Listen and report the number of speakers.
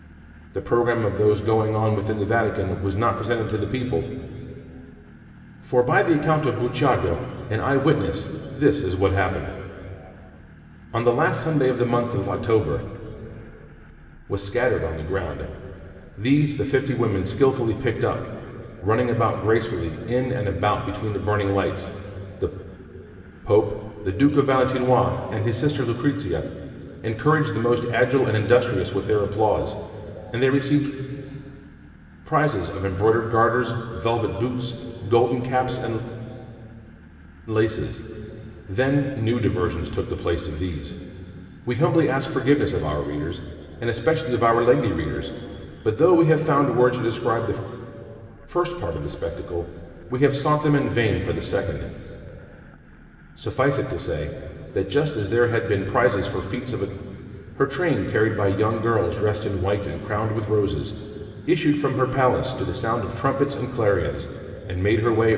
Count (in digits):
1